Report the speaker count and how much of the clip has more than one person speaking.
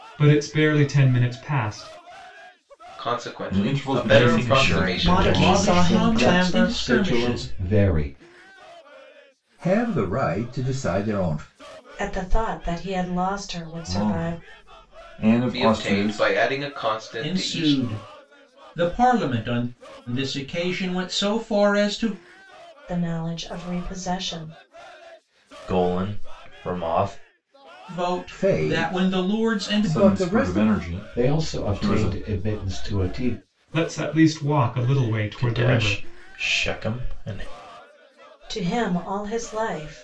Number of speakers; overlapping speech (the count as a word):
nine, about 26%